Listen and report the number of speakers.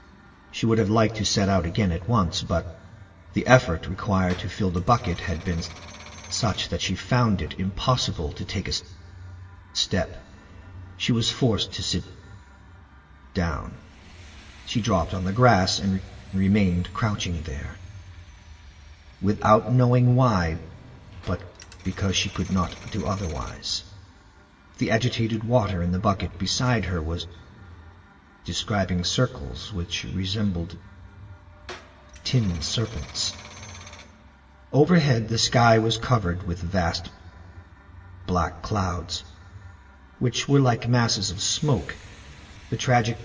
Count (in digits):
1